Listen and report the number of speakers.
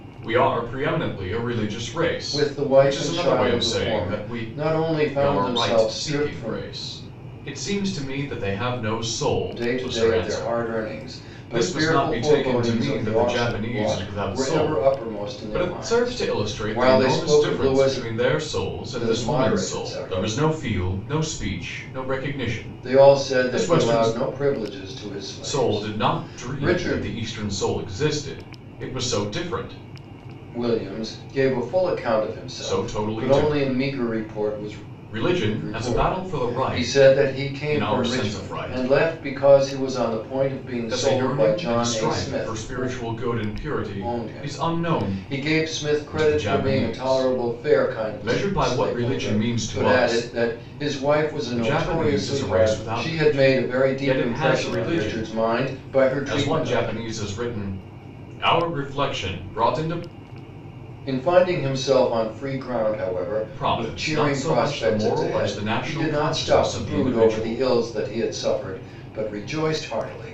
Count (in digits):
2